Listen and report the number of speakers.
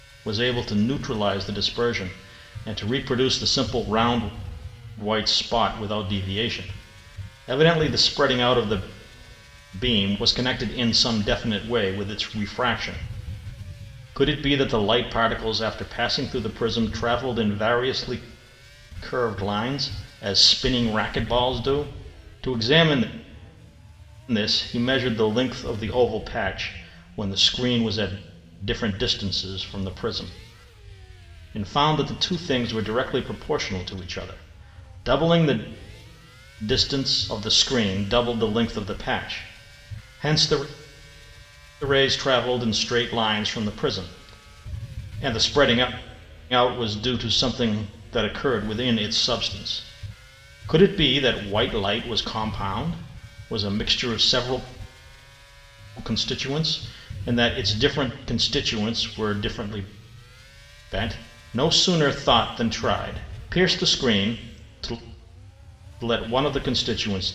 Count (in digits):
1